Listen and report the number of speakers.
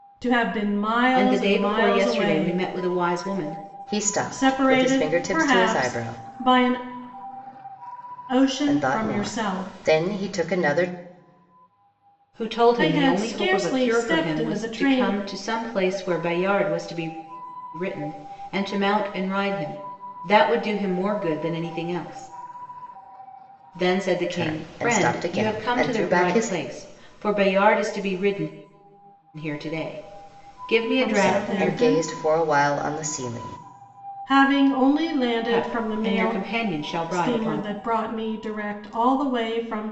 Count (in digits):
3